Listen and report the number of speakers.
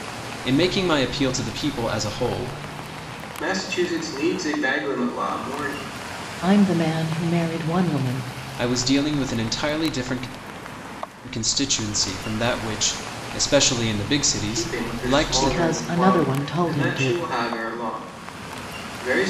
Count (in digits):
3